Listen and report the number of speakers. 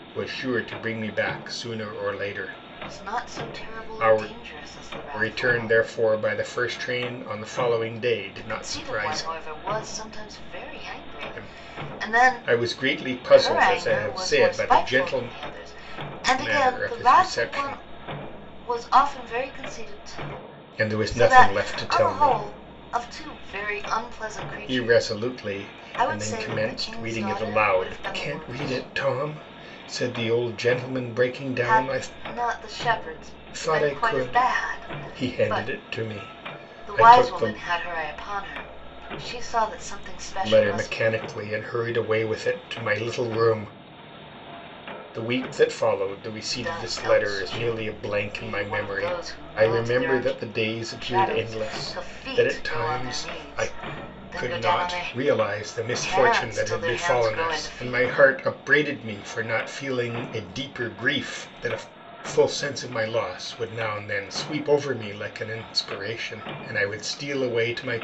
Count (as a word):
two